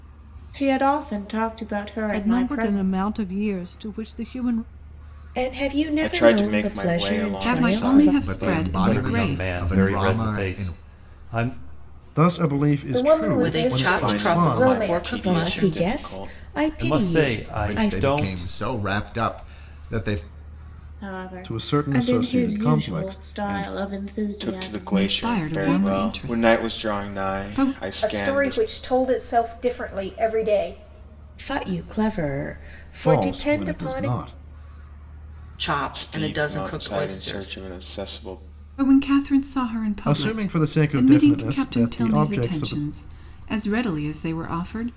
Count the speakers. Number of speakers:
10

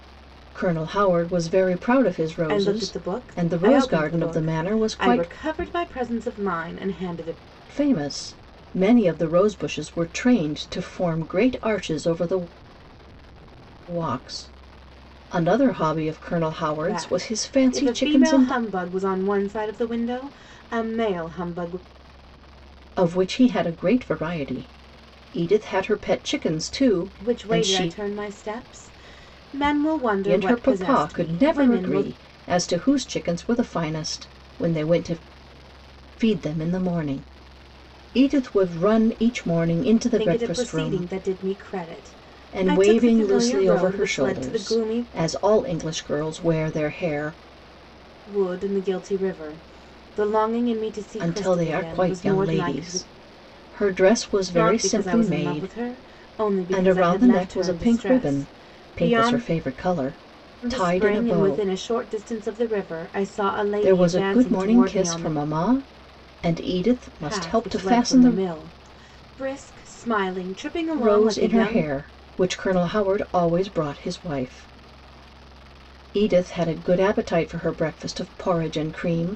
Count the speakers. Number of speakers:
2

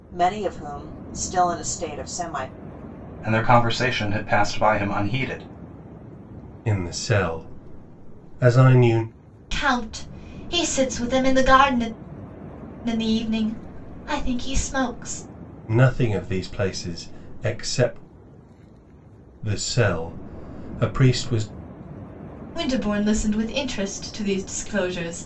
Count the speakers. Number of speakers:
4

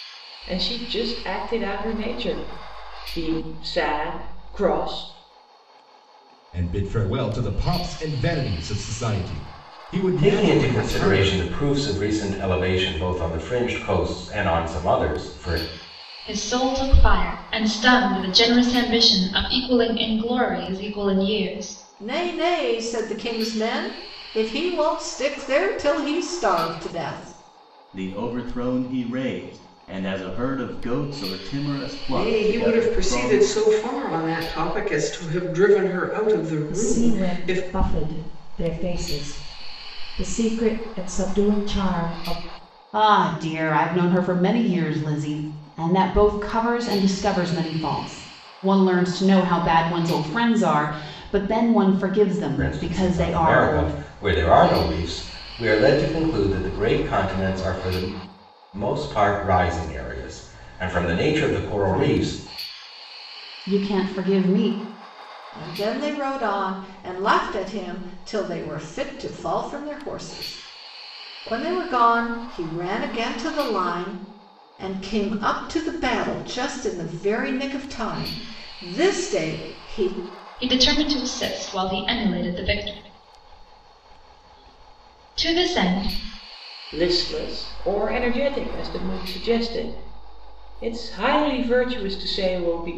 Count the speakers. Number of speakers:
9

